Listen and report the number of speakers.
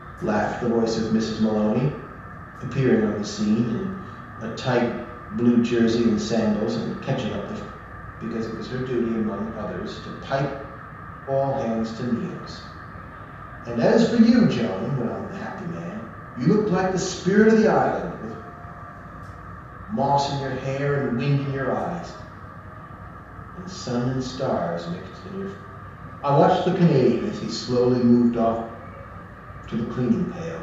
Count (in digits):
1